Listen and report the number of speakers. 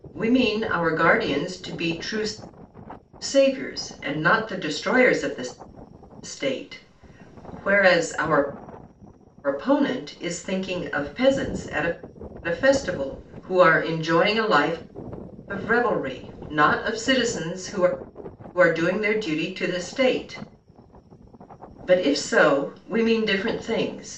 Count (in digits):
1